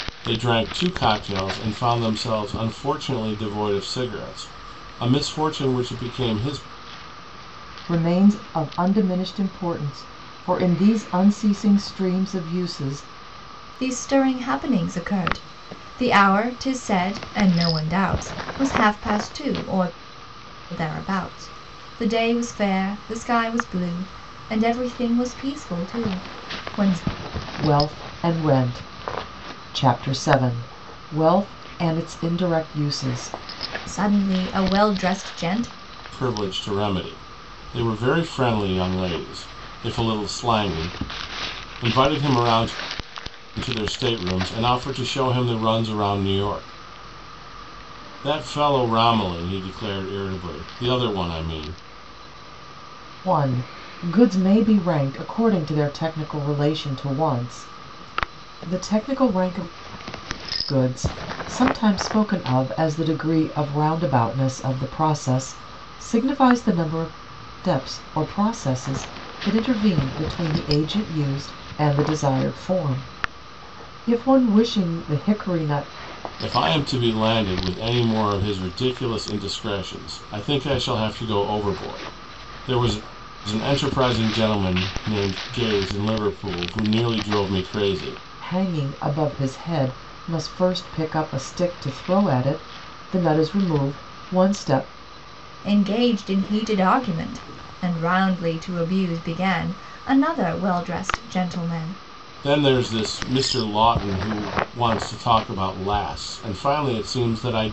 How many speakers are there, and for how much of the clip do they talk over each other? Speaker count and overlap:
3, no overlap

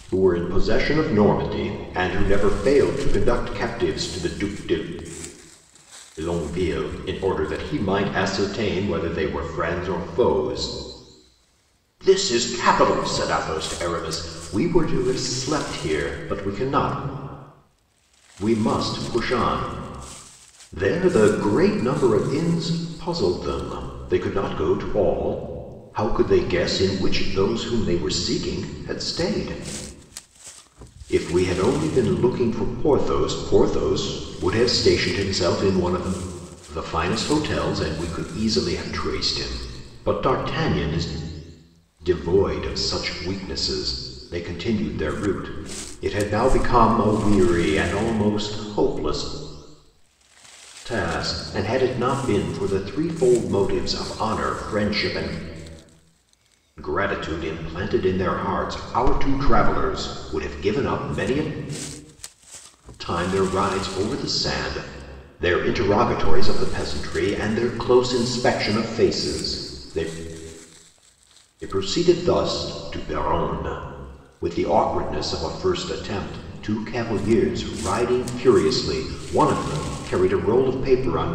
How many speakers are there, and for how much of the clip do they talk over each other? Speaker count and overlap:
1, no overlap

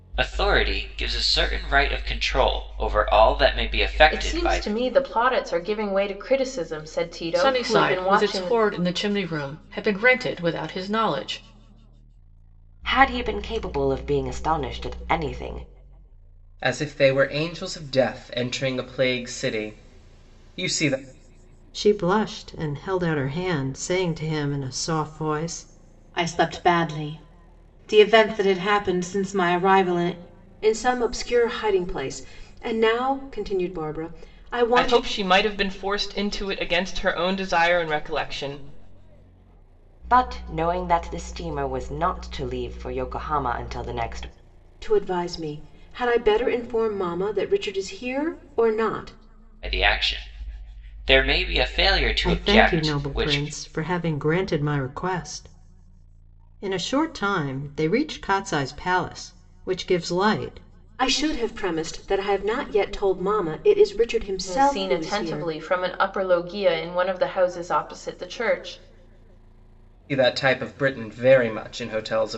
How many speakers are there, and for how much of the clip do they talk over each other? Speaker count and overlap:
9, about 6%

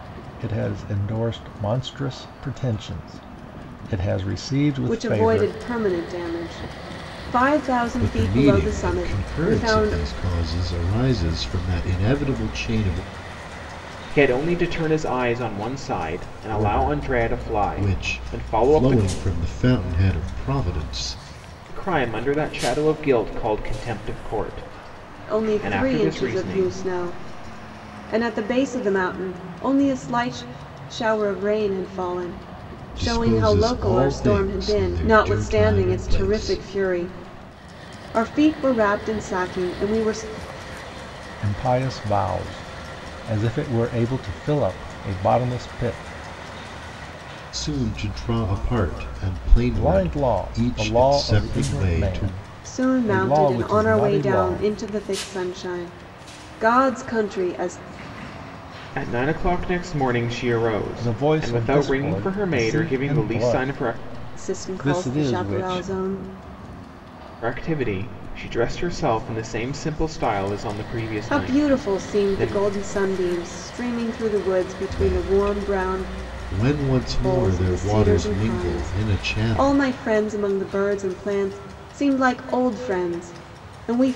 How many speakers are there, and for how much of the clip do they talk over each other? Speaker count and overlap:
4, about 30%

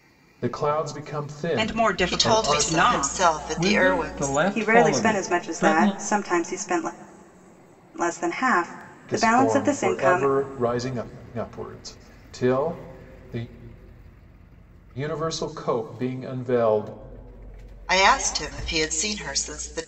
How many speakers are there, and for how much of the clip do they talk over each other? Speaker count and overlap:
5, about 26%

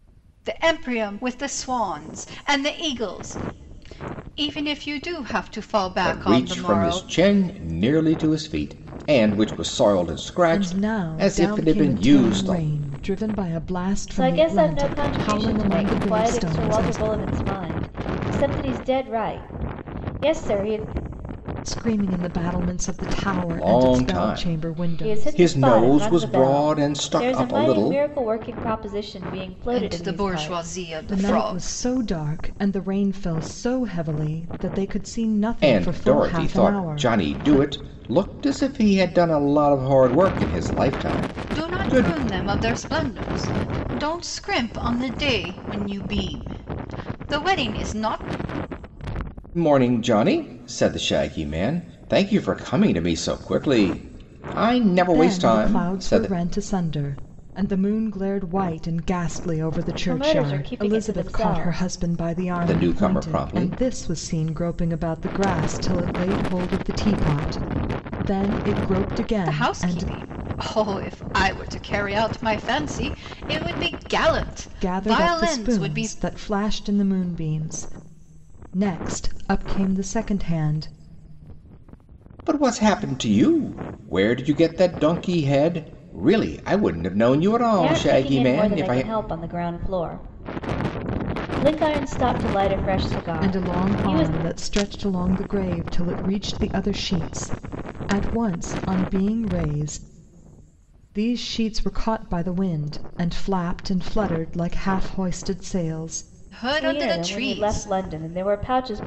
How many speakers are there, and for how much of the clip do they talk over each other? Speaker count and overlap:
4, about 23%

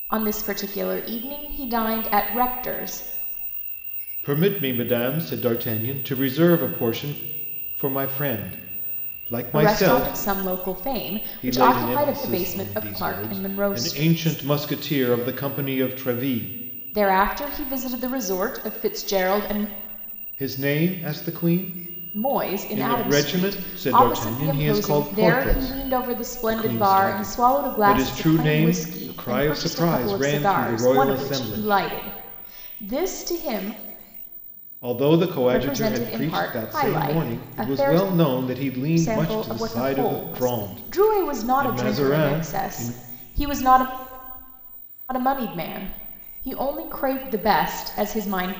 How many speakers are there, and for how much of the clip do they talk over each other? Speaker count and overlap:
2, about 39%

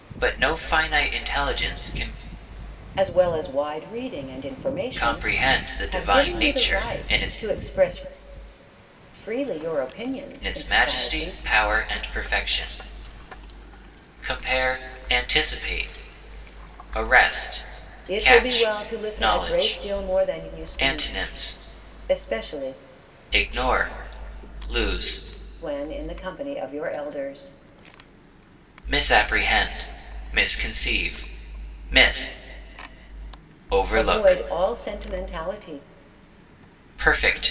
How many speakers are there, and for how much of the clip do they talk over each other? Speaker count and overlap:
2, about 17%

